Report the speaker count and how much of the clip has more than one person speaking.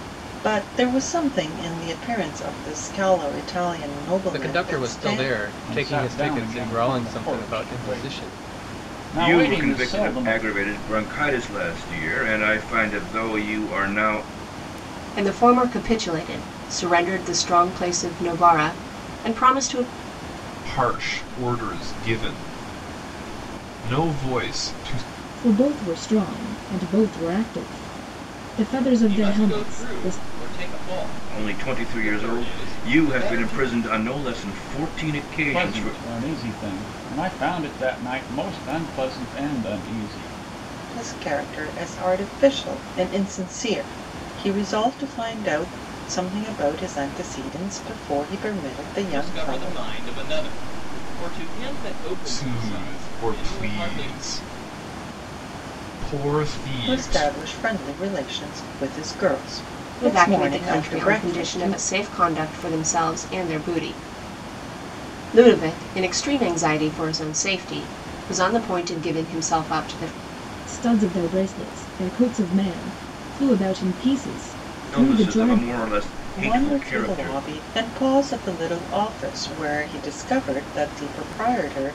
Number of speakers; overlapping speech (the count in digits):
8, about 20%